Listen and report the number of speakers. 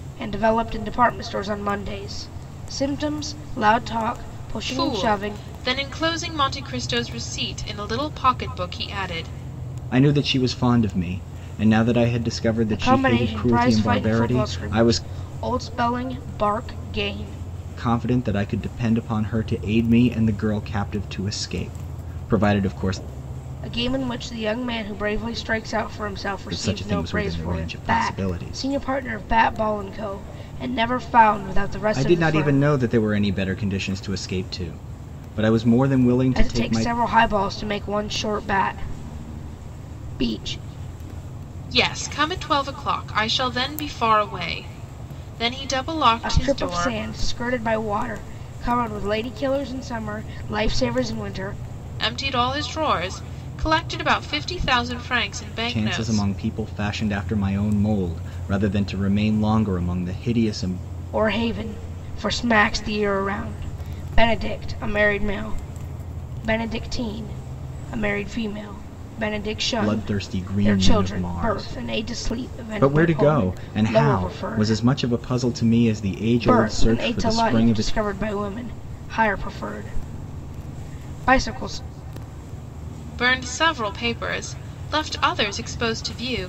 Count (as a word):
three